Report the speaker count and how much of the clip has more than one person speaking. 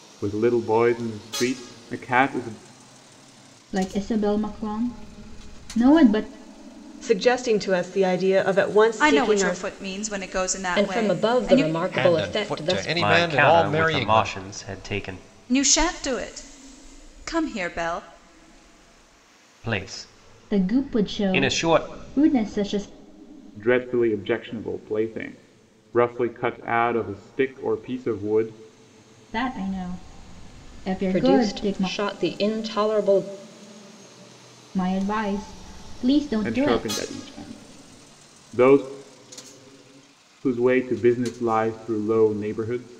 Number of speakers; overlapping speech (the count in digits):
7, about 16%